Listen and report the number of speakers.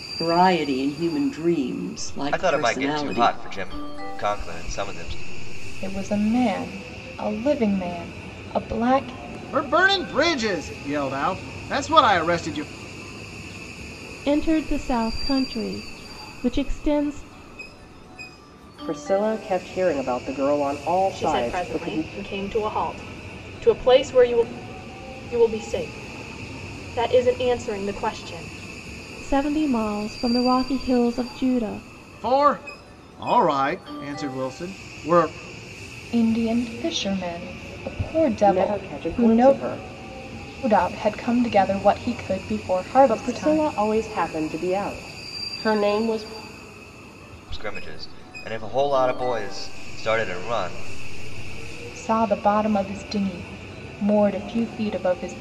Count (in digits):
7